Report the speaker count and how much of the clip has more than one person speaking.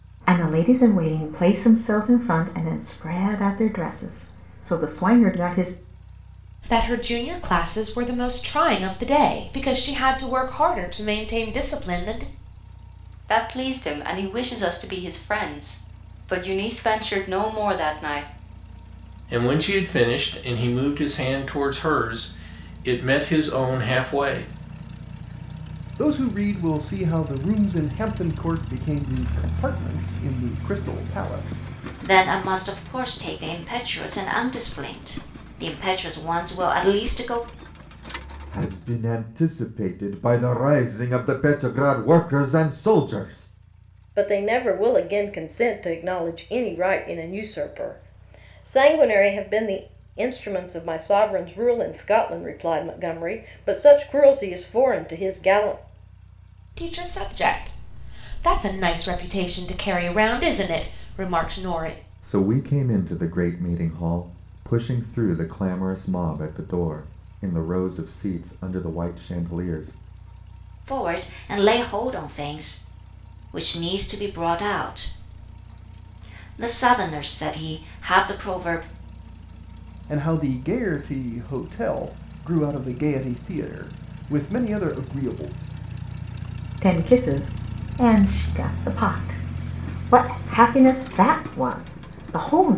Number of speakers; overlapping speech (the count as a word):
eight, no overlap